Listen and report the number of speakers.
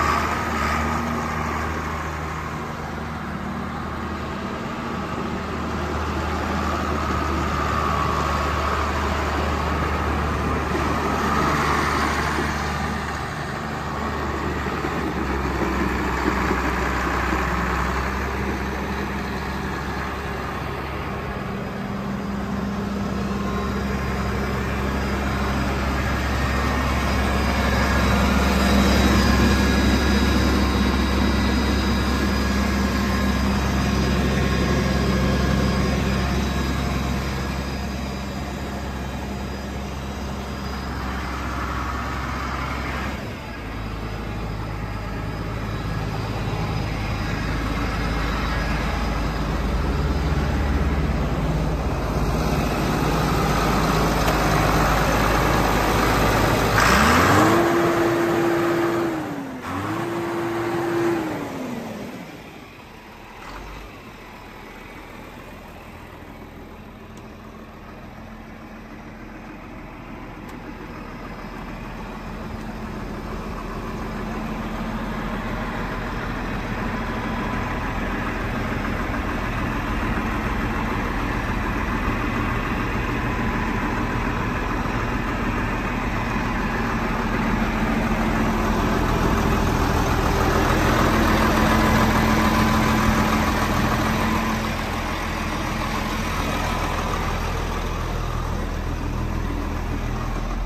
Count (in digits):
0